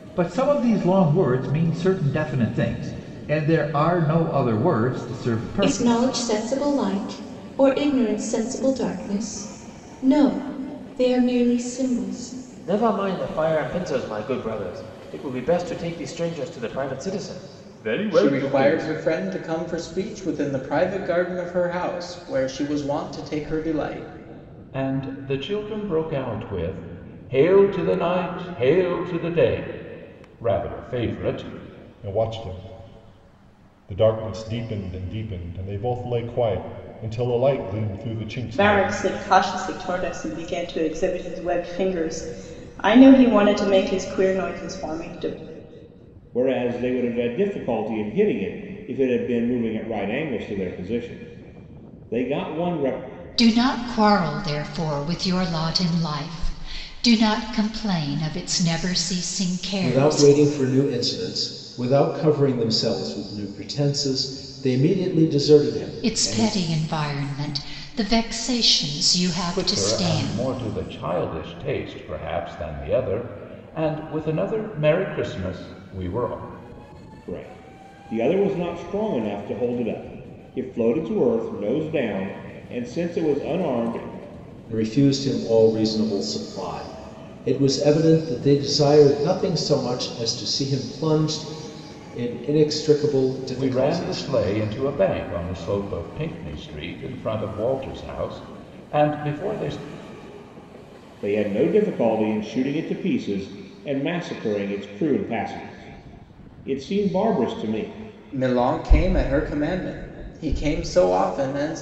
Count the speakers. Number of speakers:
10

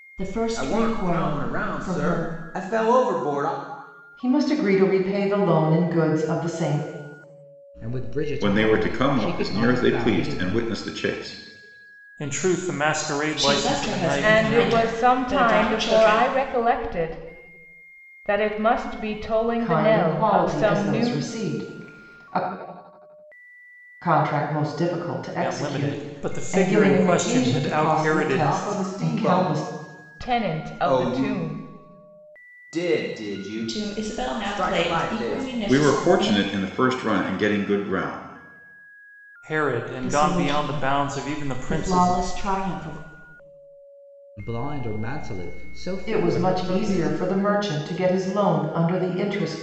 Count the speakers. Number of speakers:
8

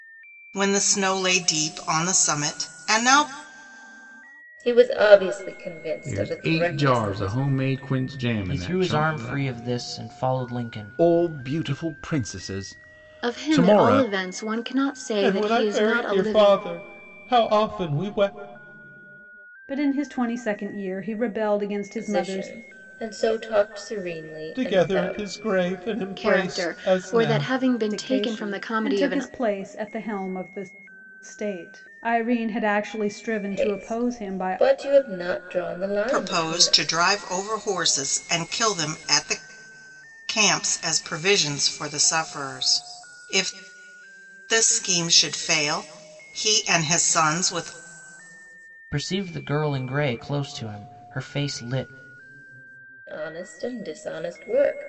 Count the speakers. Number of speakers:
8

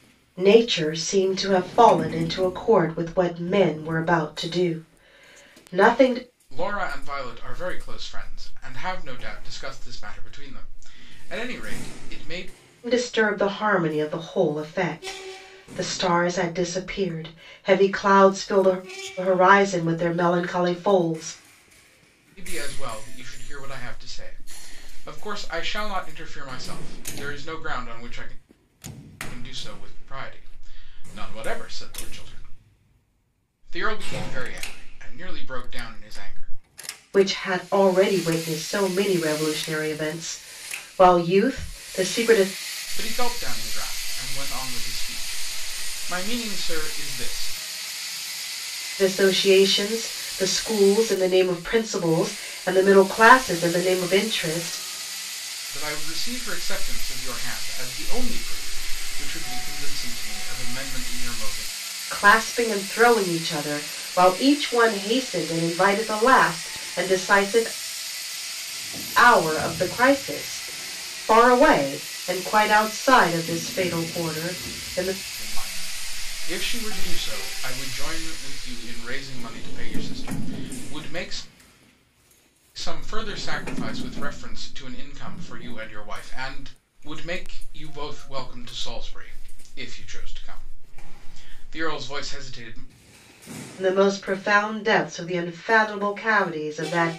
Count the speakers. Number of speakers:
2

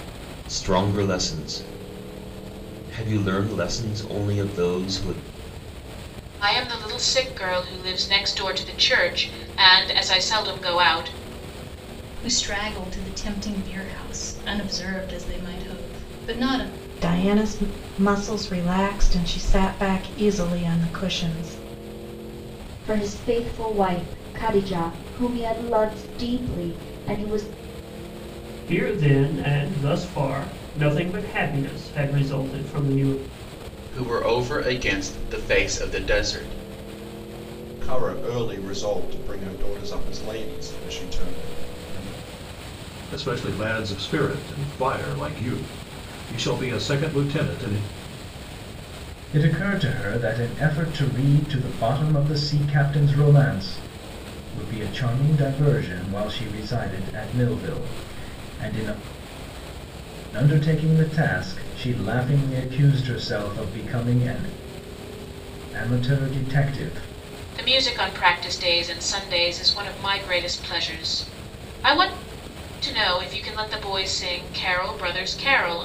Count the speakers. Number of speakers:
10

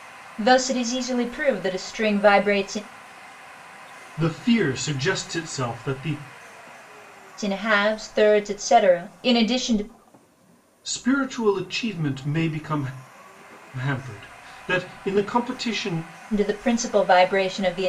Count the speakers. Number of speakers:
2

